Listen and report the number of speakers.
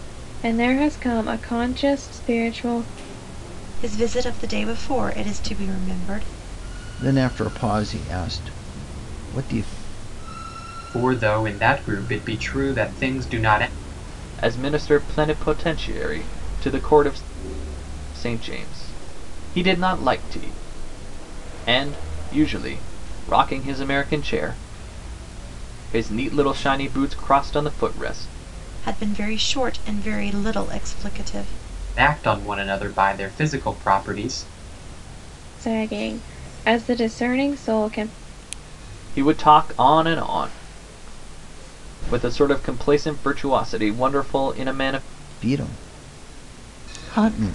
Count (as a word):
five